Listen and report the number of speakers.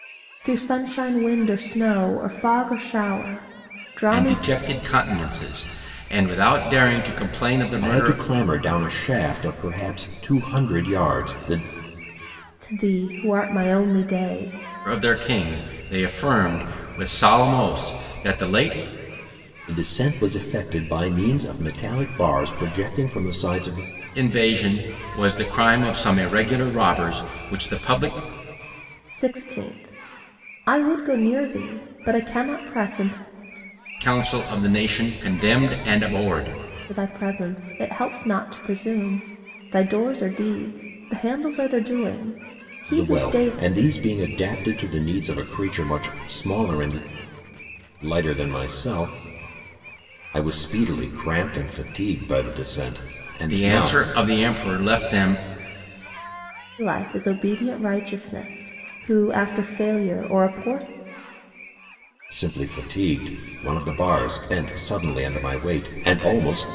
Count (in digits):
3